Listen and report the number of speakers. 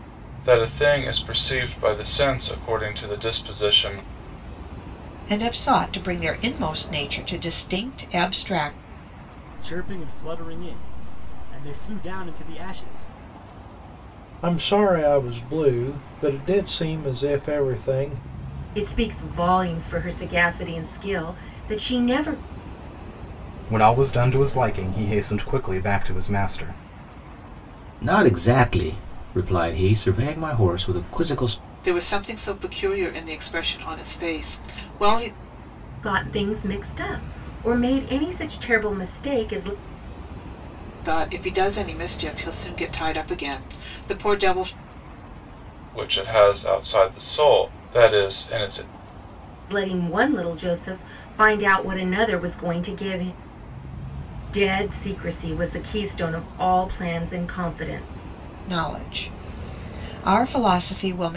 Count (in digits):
8